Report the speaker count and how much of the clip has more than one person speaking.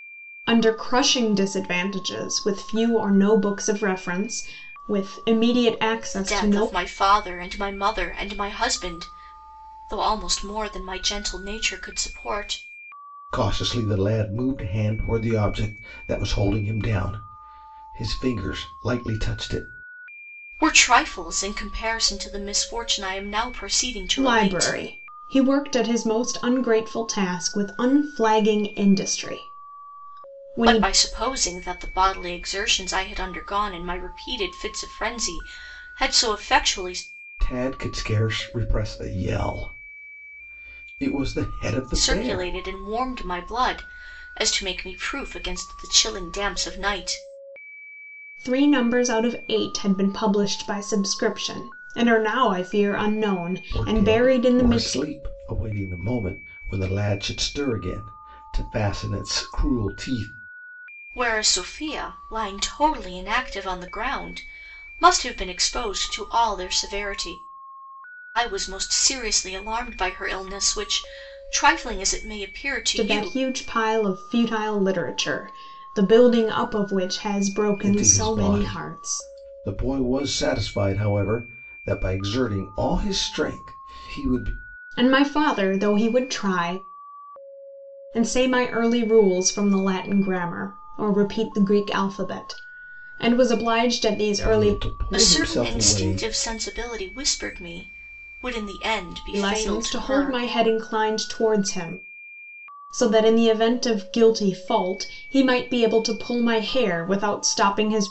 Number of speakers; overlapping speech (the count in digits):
3, about 7%